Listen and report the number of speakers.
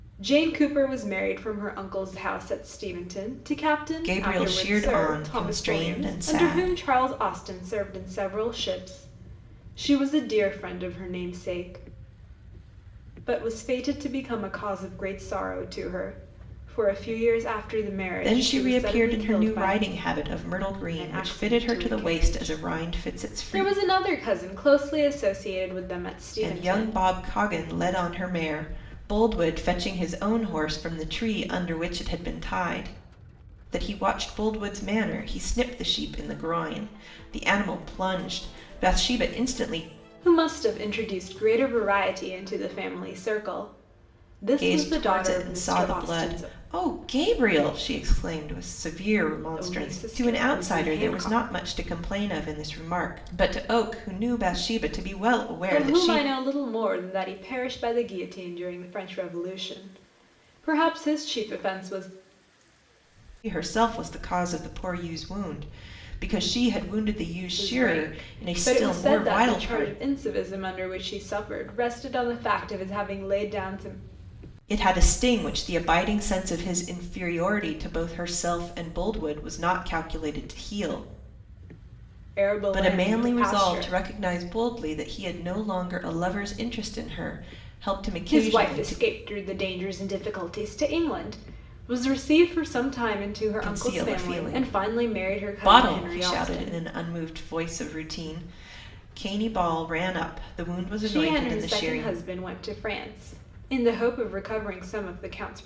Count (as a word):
two